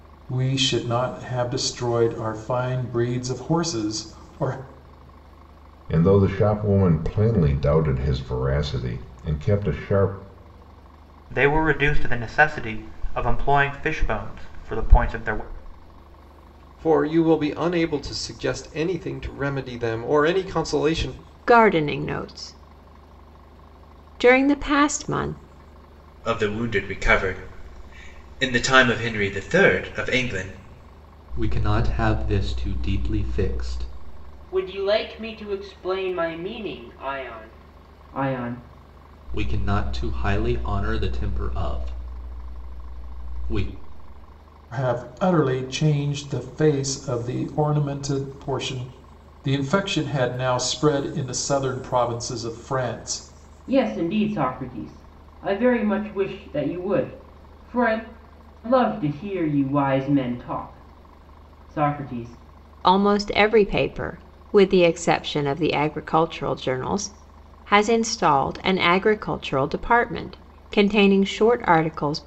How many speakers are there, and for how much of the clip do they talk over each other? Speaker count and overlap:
eight, no overlap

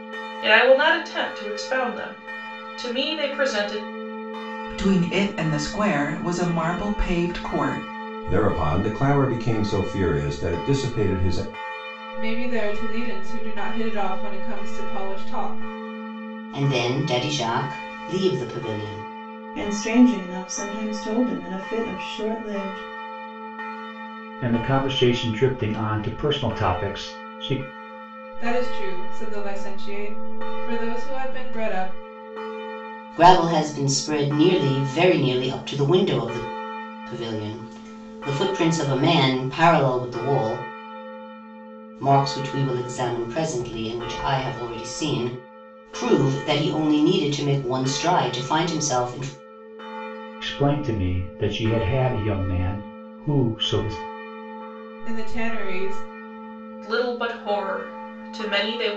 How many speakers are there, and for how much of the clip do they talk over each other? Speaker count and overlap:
seven, no overlap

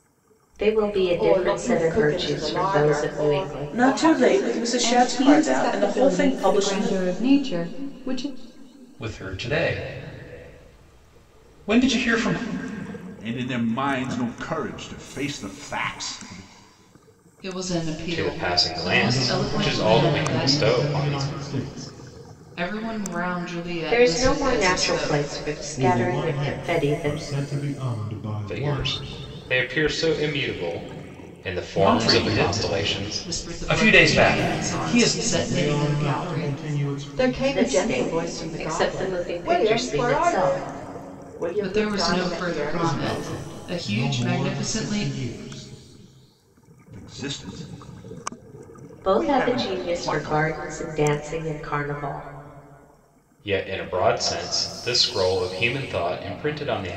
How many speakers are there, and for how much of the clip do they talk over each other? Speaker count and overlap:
nine, about 46%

